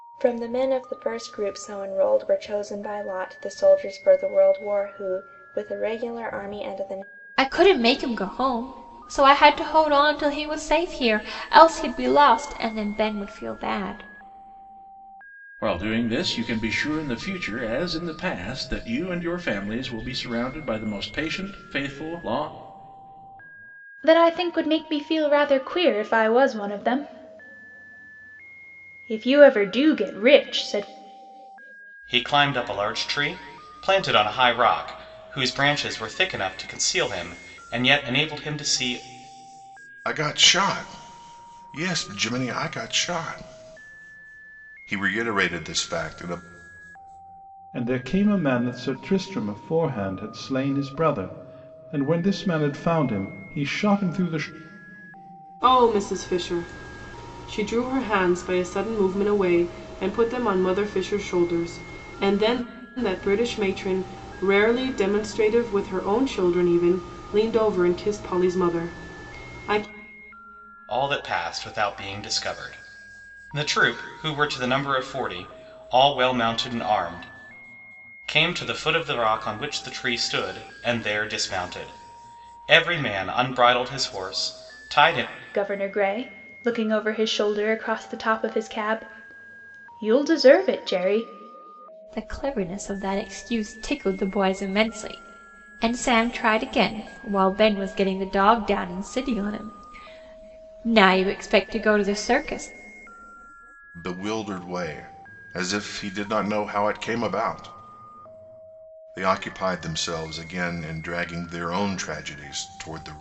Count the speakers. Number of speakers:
eight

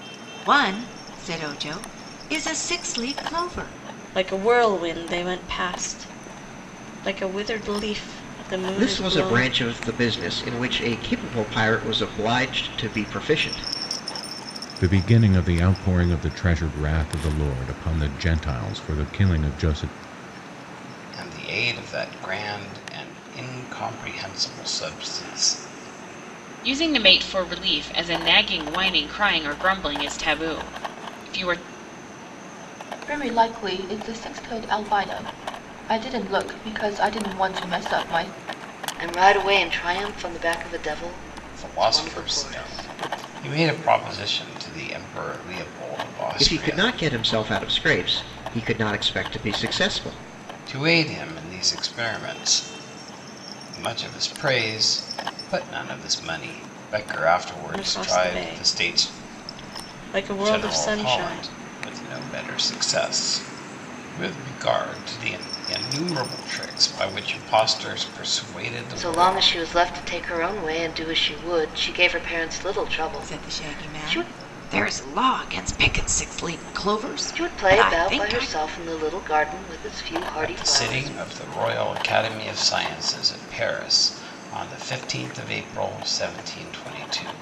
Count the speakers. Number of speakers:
eight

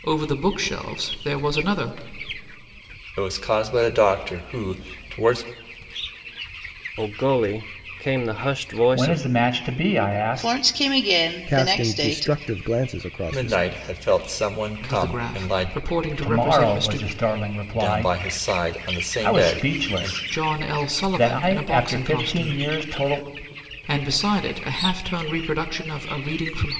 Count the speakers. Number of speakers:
six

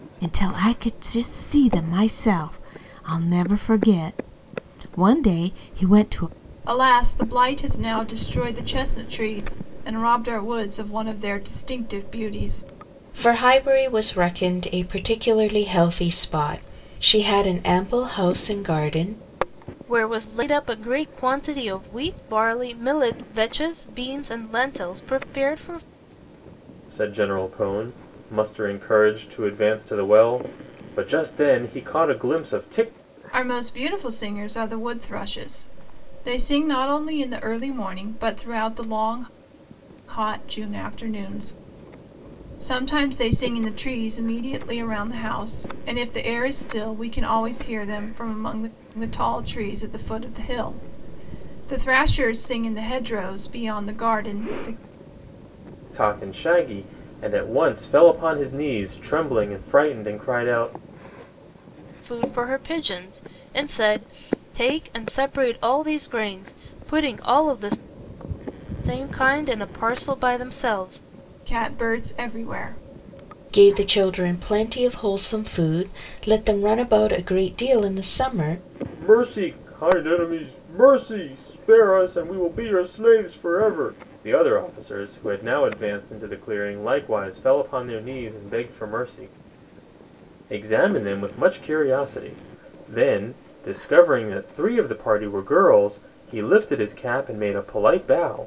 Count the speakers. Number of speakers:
five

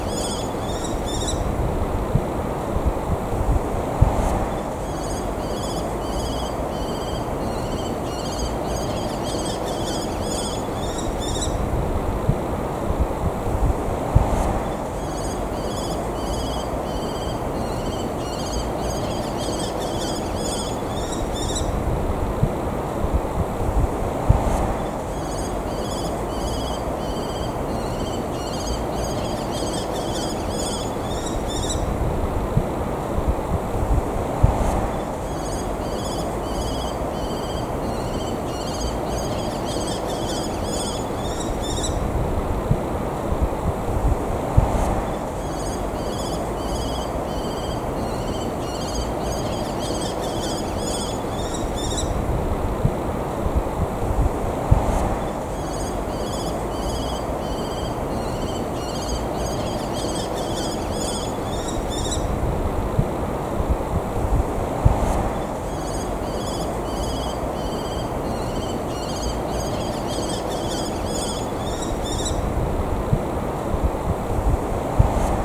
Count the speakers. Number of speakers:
zero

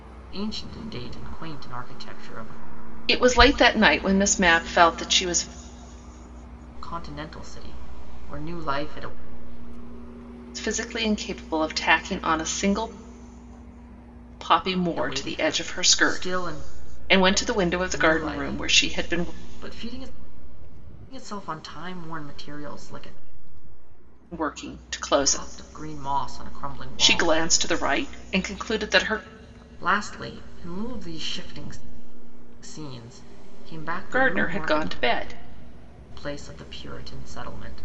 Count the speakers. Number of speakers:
two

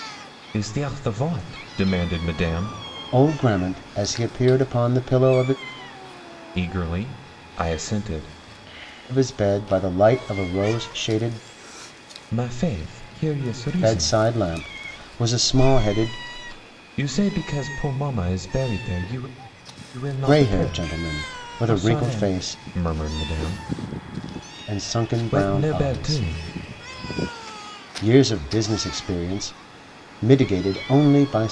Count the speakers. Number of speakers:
two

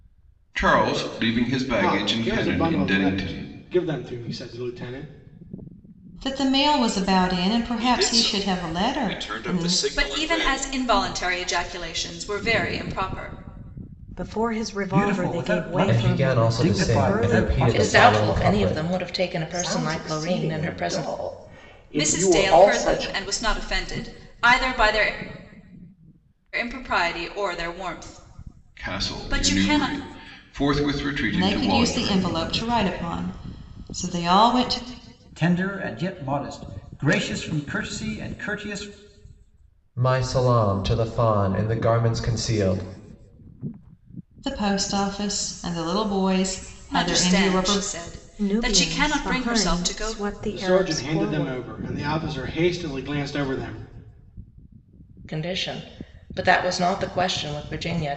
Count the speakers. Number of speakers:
ten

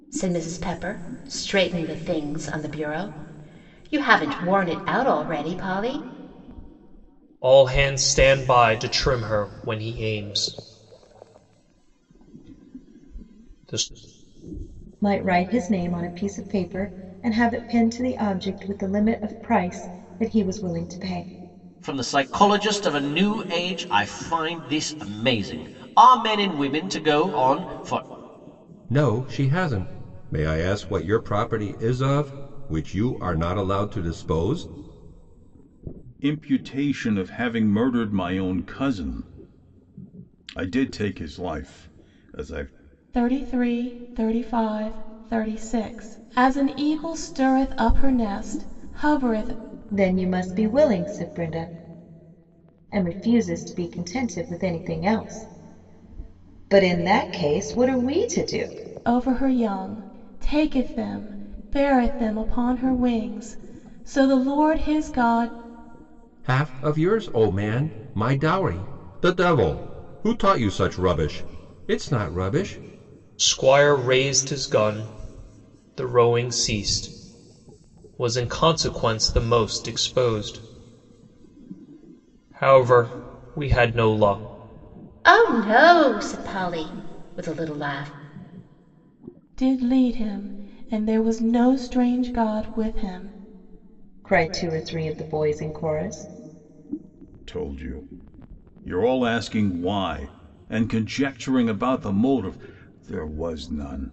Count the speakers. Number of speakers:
seven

